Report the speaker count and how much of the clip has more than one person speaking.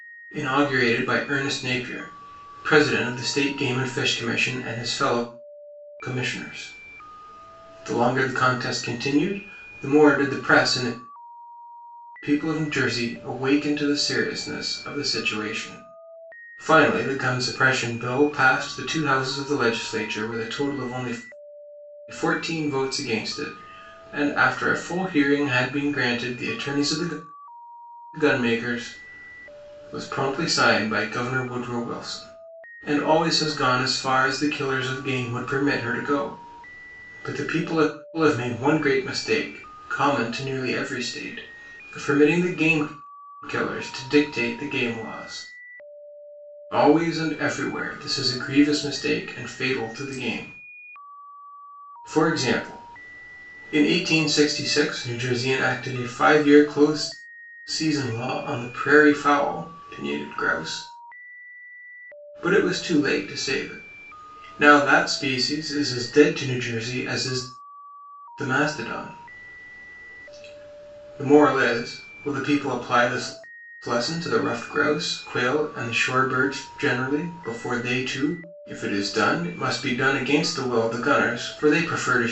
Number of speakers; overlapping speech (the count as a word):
one, no overlap